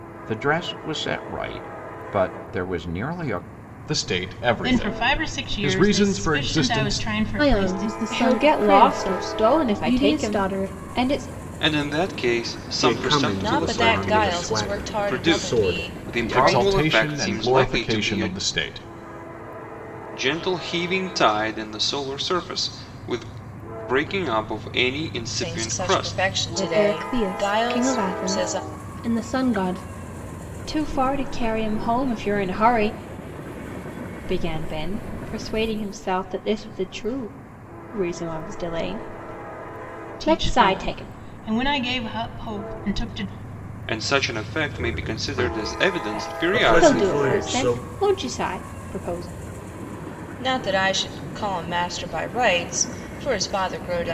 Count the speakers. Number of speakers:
8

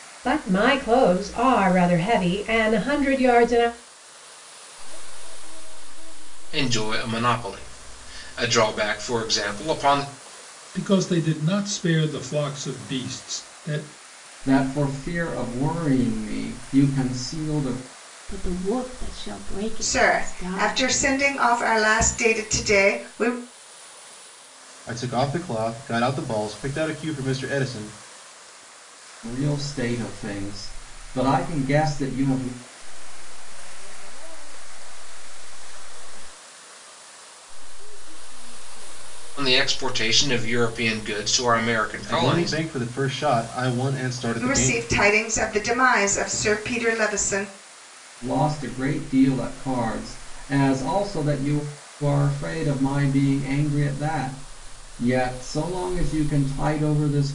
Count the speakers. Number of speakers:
8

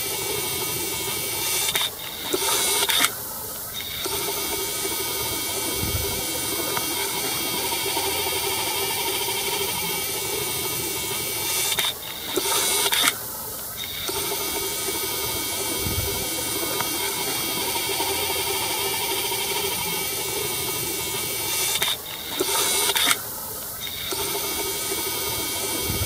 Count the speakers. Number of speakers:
0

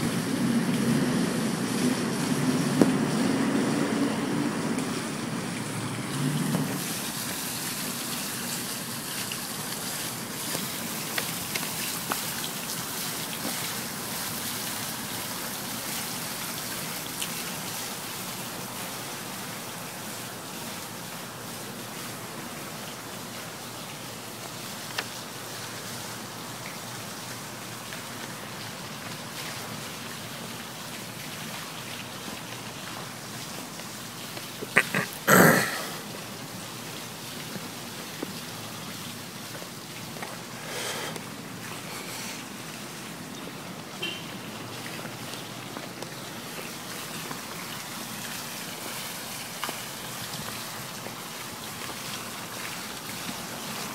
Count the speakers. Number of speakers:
0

